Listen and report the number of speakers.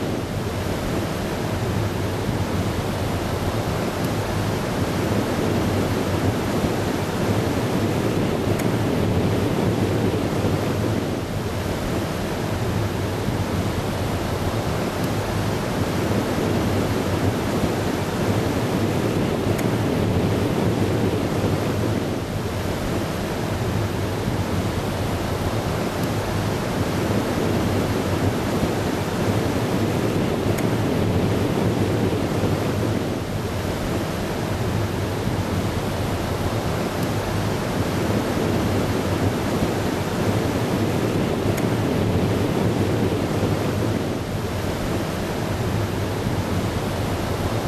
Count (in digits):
0